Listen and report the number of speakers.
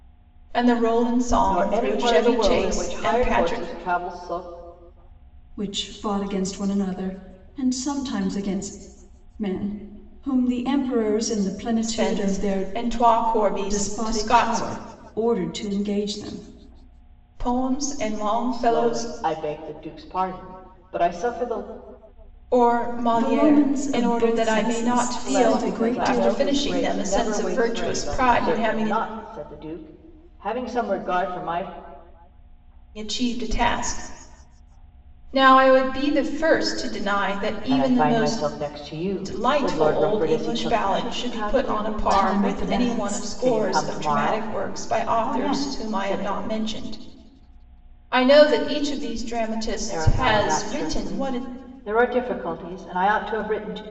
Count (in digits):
3